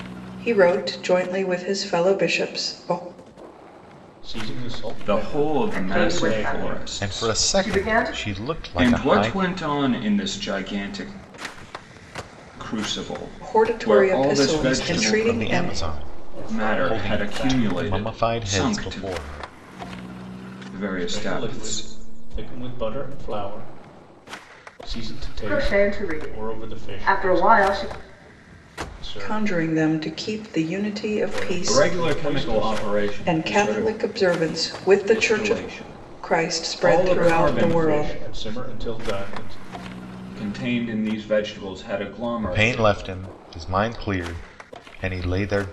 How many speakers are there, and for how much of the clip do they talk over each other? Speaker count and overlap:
5, about 42%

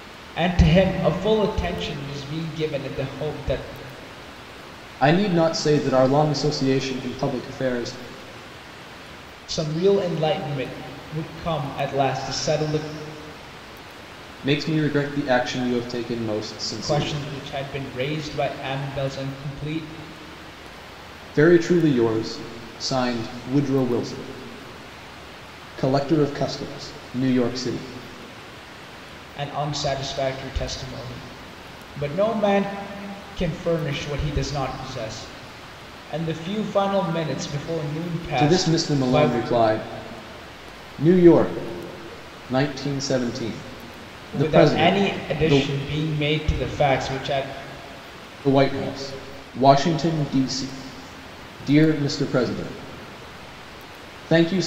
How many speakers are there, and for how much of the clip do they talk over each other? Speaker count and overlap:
2, about 5%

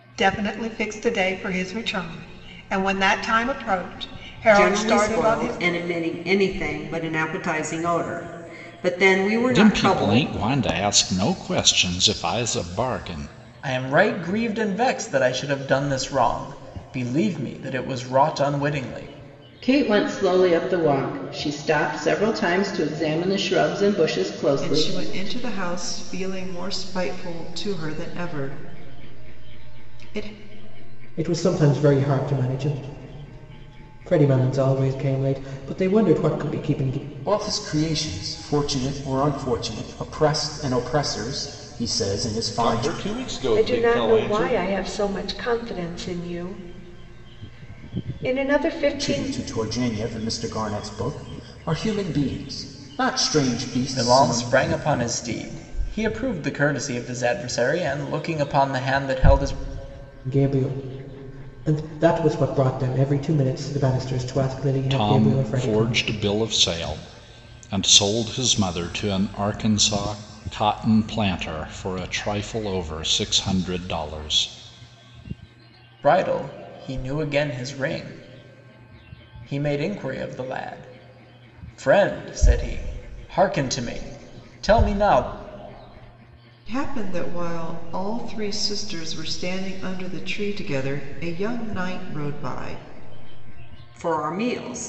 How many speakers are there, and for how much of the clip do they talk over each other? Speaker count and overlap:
10, about 7%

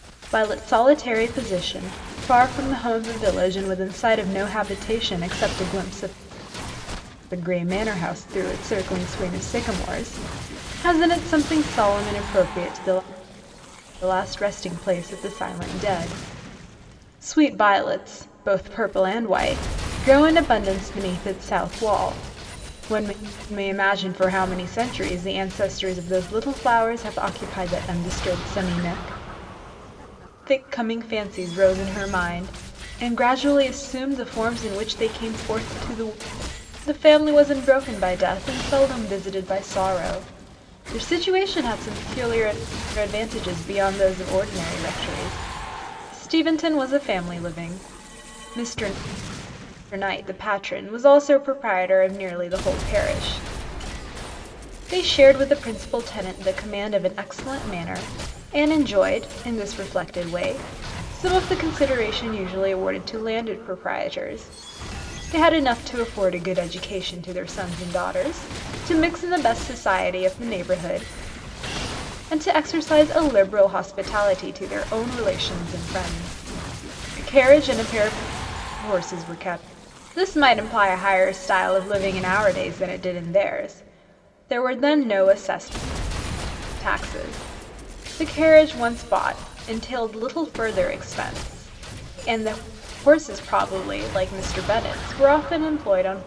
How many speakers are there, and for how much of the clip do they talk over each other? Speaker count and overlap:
1, no overlap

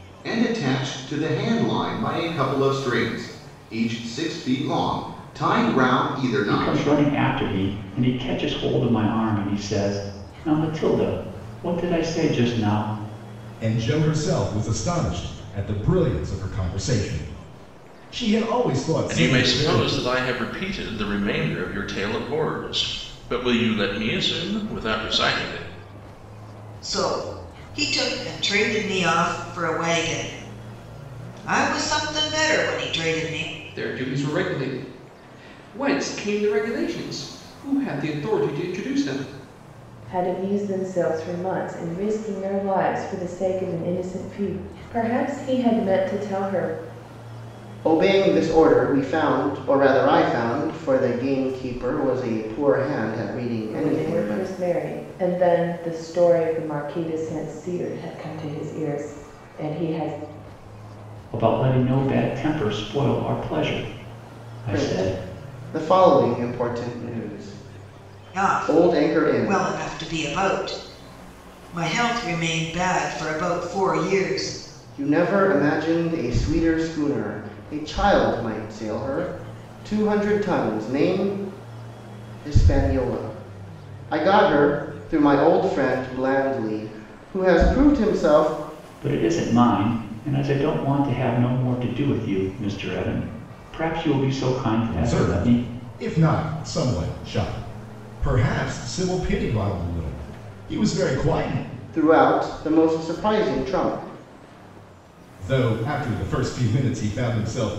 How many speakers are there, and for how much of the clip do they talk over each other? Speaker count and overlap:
8, about 4%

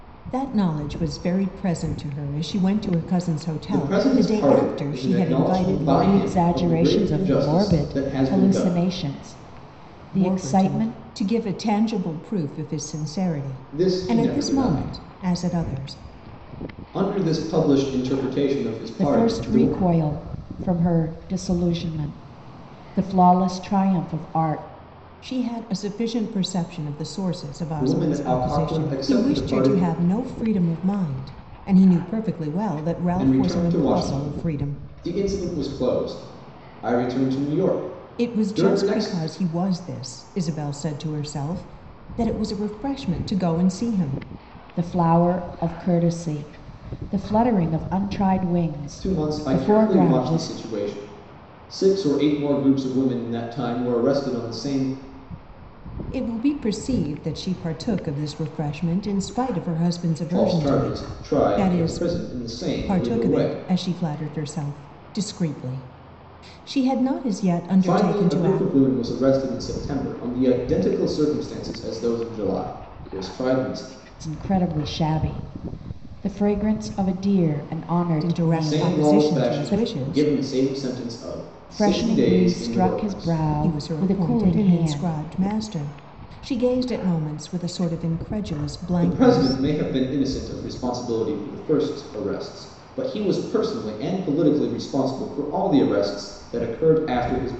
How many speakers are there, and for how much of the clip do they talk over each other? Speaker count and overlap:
3, about 26%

